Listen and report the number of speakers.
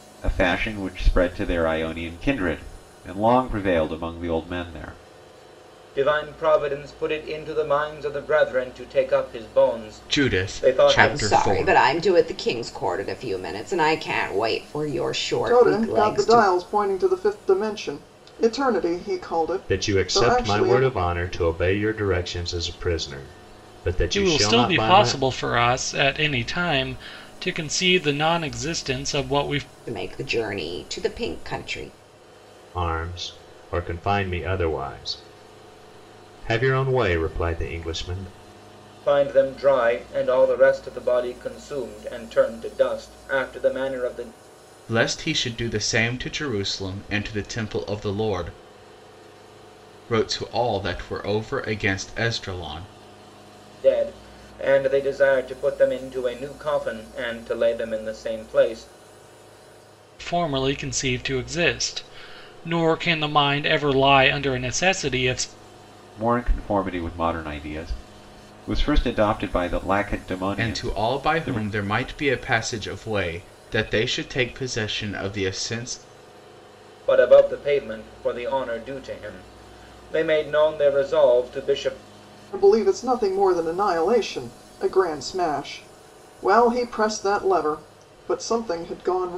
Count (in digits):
7